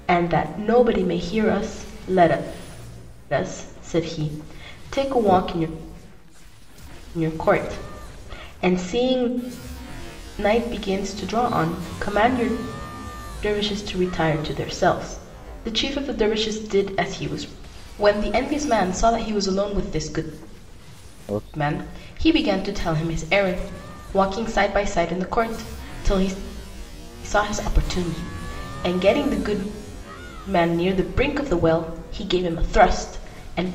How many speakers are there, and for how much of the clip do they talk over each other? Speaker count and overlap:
1, no overlap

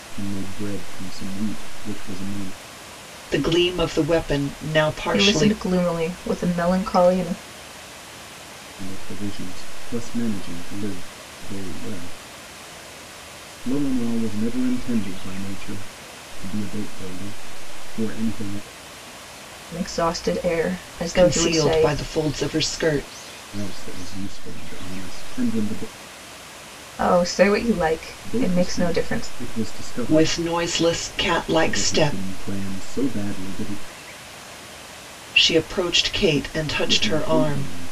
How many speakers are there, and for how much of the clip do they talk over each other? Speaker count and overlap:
3, about 12%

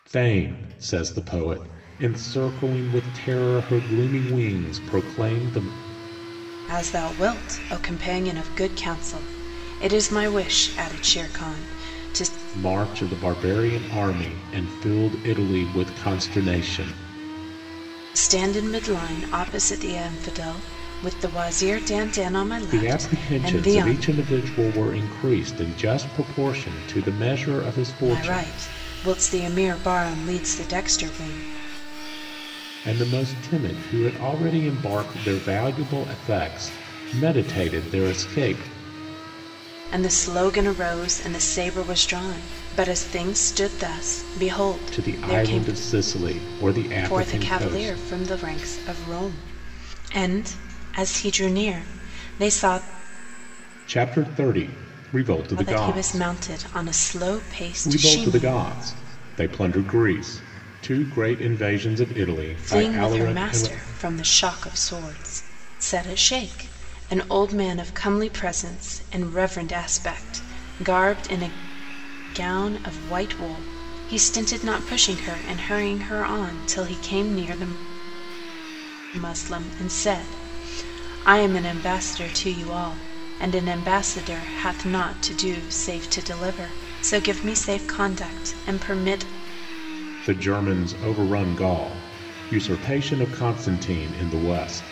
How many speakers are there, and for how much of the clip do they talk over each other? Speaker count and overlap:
2, about 7%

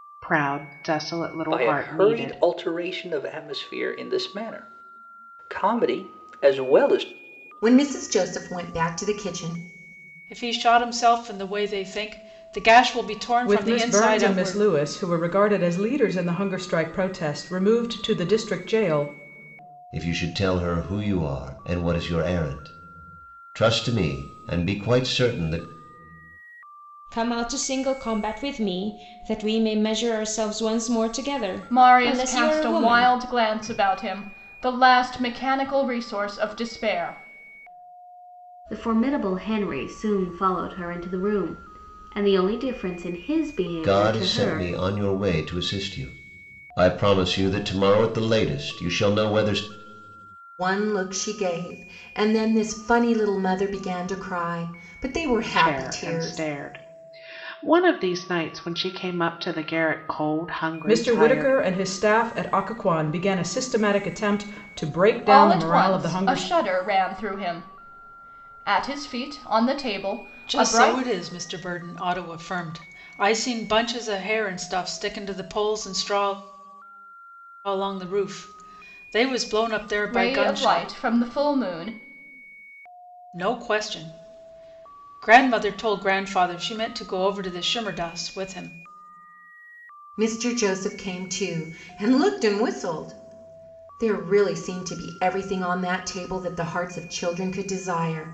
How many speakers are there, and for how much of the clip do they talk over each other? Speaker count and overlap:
9, about 9%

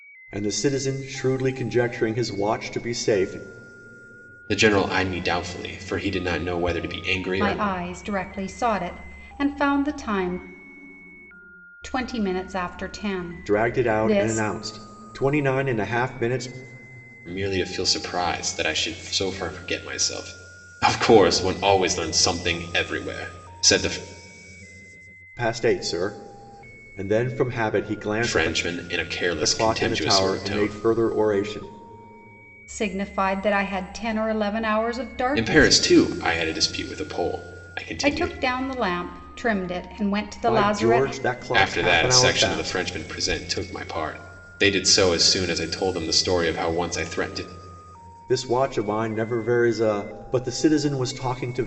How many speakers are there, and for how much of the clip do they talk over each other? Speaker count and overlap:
3, about 12%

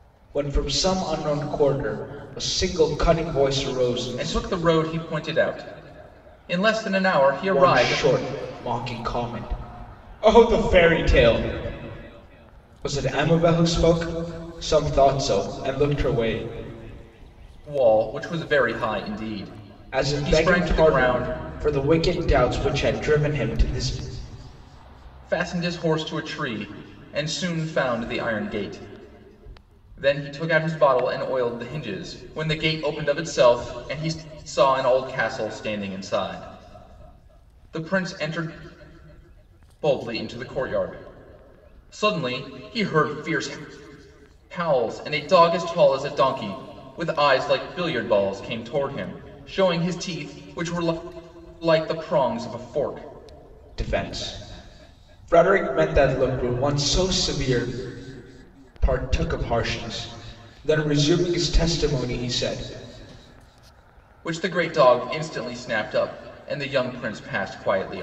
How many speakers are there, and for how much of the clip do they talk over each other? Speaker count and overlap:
2, about 4%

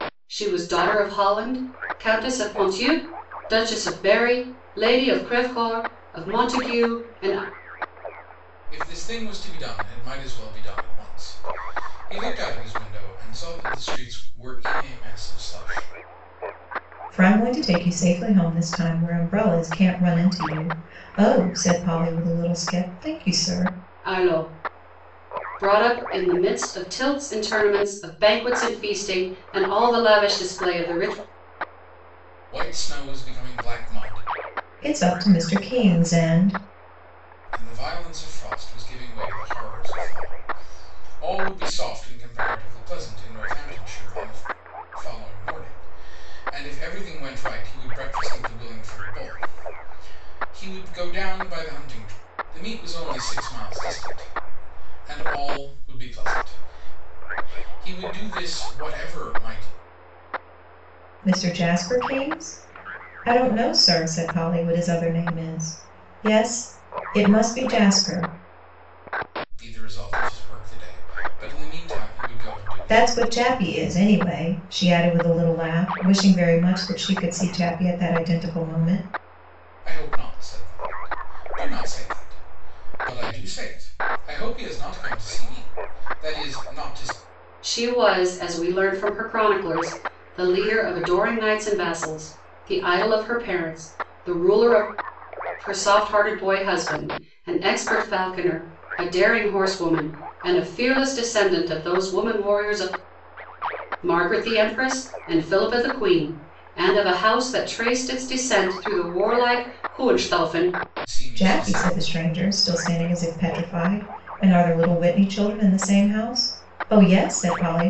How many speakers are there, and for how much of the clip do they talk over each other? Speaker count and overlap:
3, about 1%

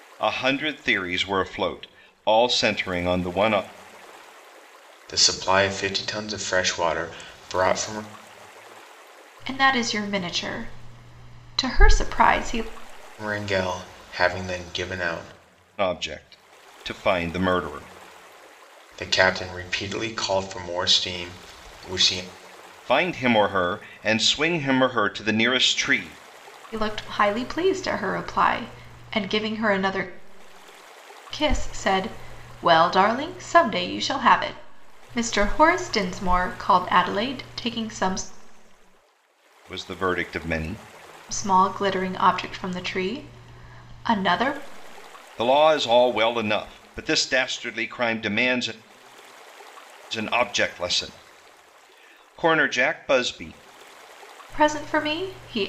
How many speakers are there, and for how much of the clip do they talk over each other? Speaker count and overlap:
3, no overlap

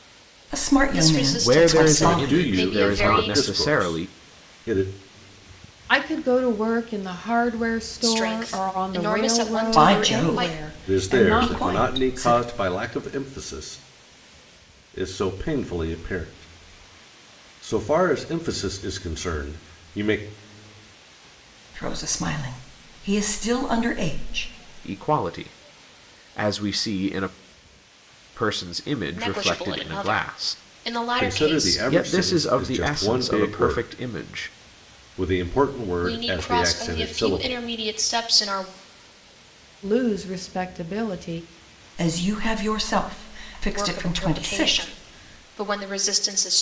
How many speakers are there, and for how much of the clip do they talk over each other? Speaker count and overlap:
5, about 32%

